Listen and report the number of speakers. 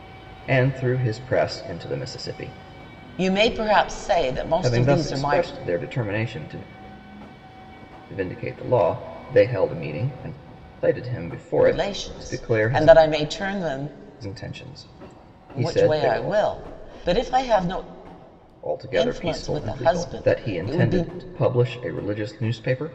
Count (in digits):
2